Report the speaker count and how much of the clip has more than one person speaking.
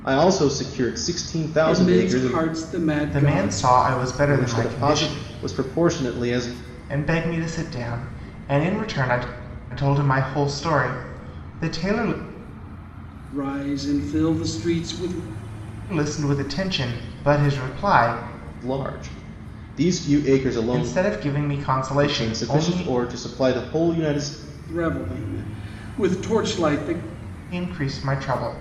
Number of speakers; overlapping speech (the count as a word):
three, about 13%